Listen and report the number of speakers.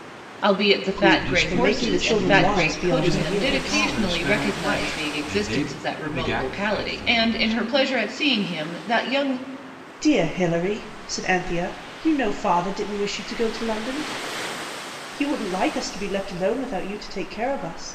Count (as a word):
three